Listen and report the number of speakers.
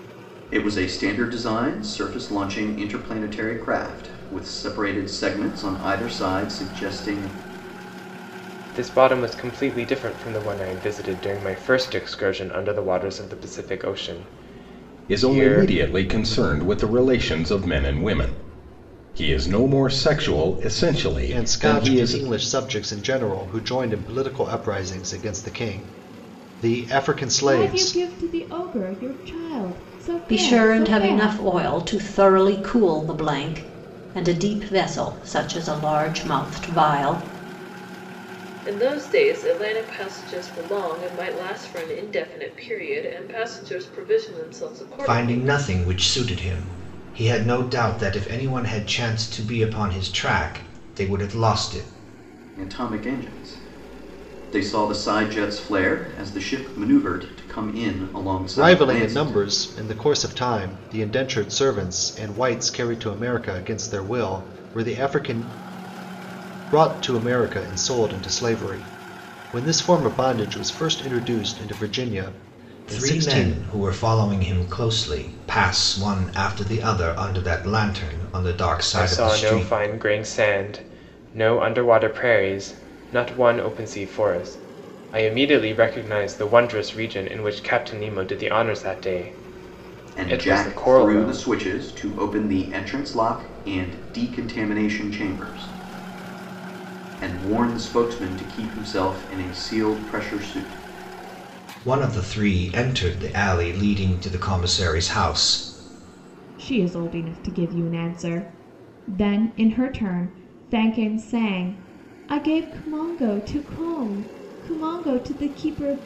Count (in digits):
8